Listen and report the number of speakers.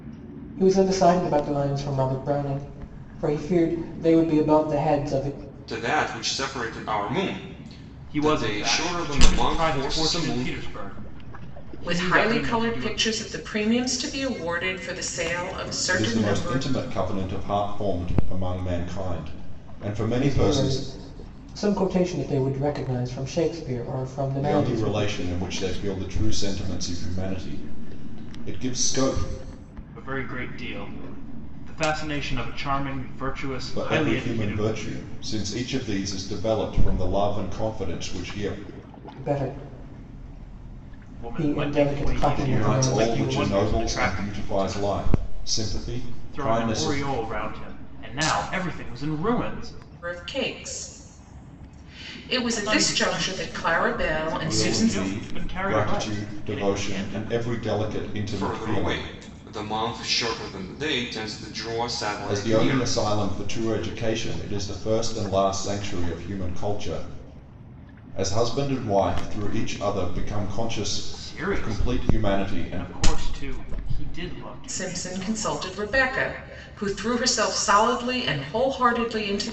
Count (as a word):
five